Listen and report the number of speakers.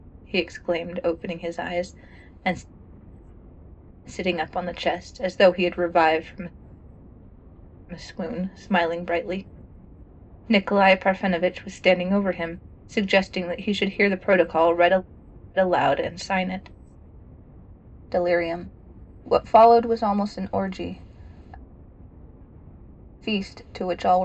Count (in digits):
1